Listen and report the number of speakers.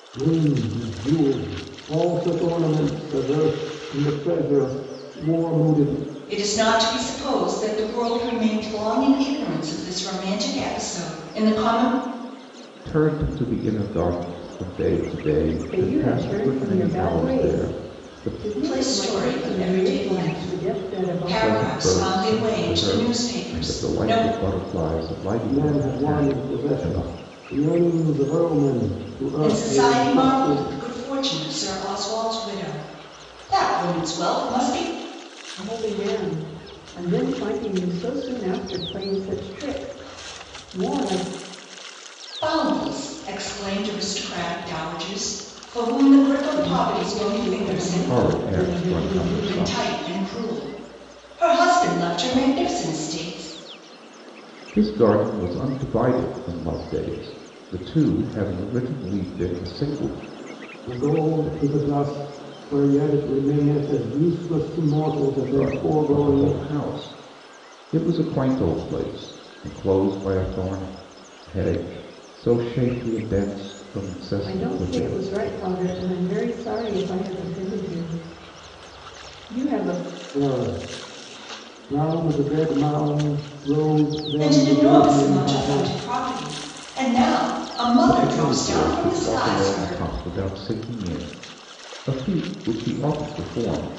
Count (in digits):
4